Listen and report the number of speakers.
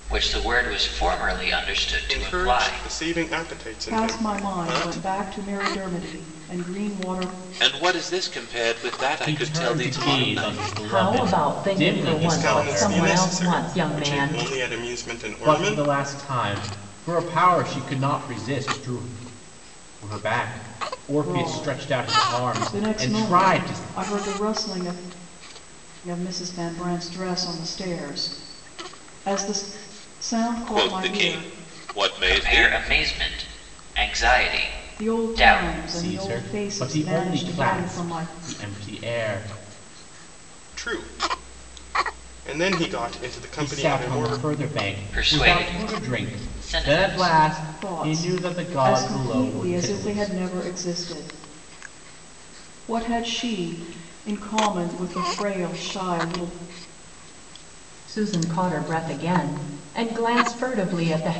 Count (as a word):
six